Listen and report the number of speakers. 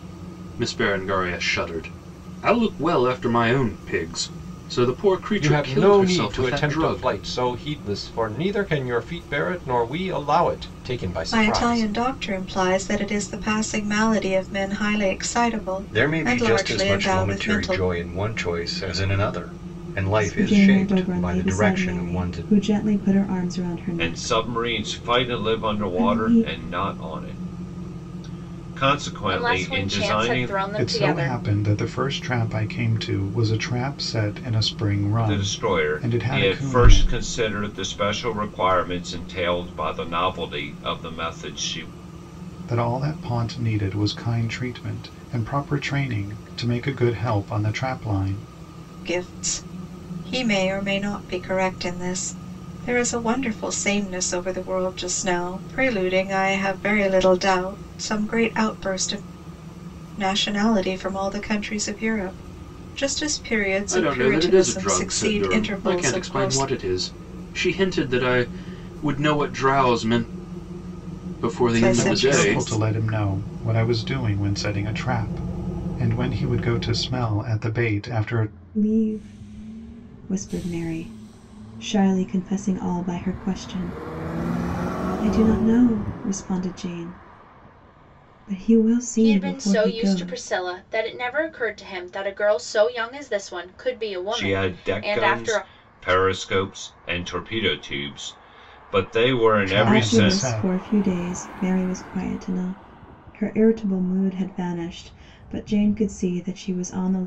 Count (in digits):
8